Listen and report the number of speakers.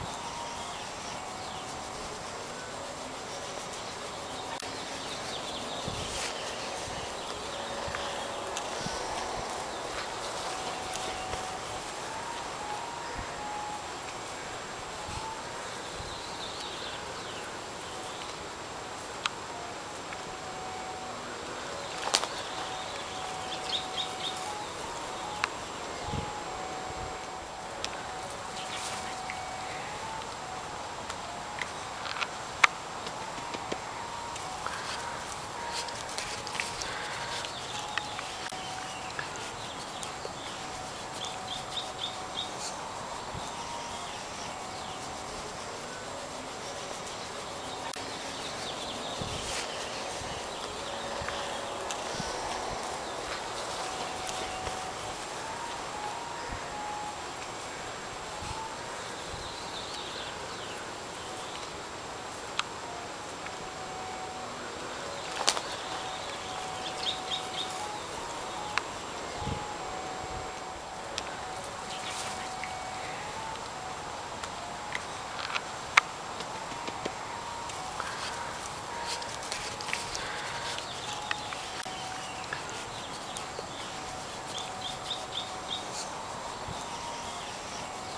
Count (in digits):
0